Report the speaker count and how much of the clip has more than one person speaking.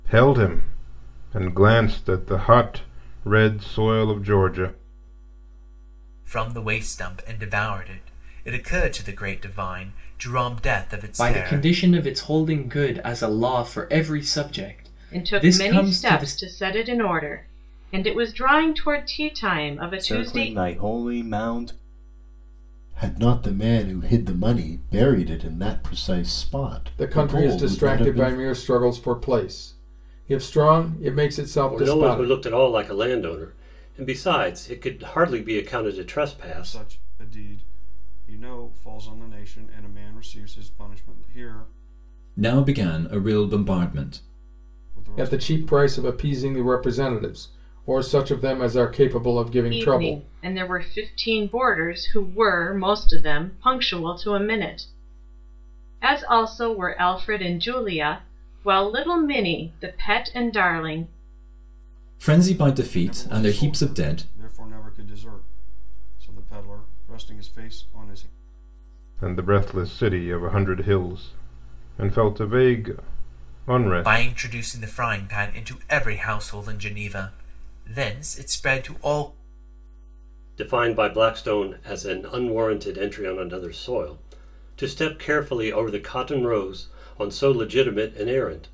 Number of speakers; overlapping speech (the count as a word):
ten, about 9%